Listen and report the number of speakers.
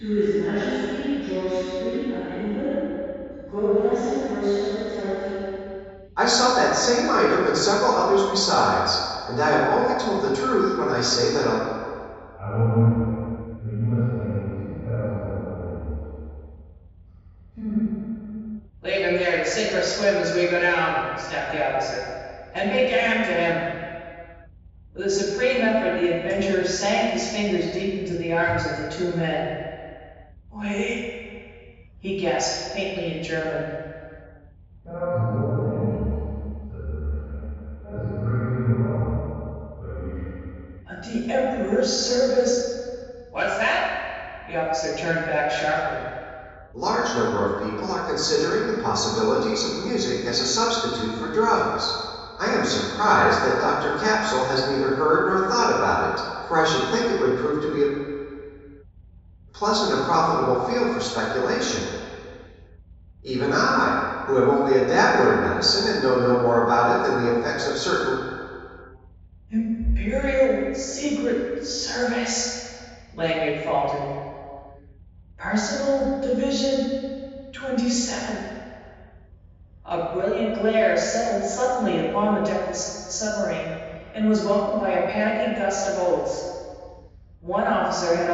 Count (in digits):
4